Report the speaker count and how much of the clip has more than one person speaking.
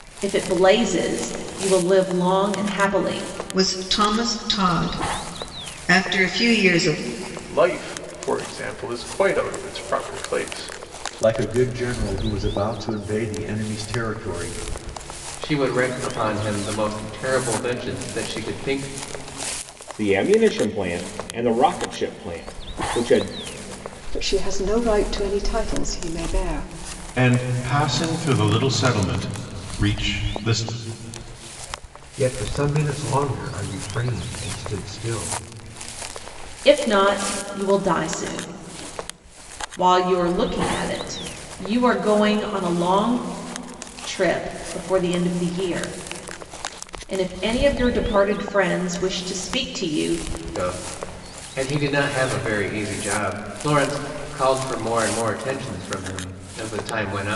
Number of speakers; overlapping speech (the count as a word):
nine, no overlap